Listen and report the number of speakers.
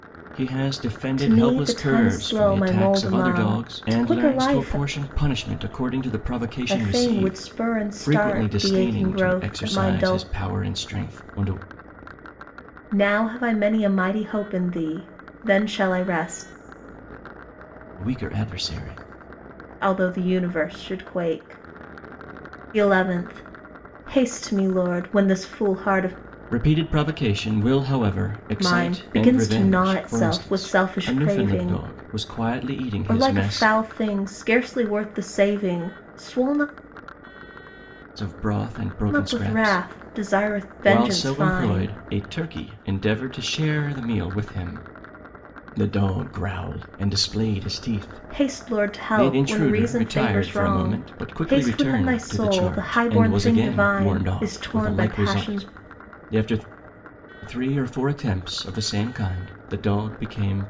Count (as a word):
two